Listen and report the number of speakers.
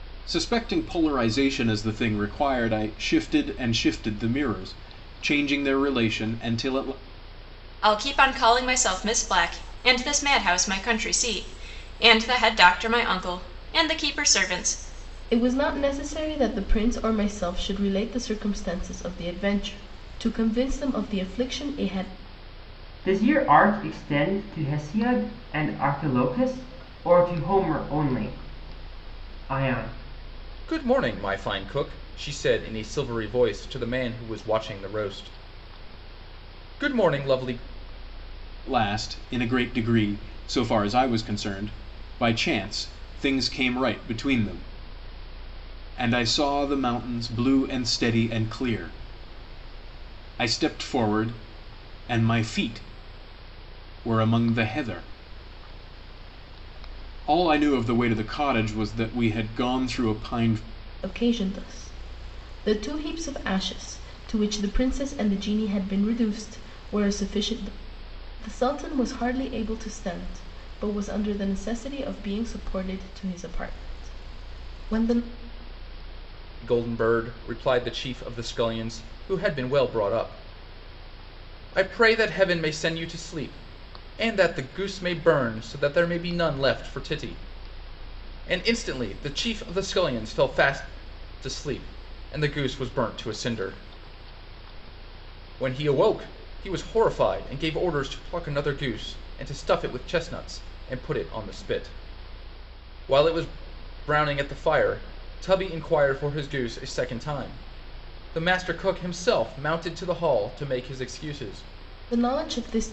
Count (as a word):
five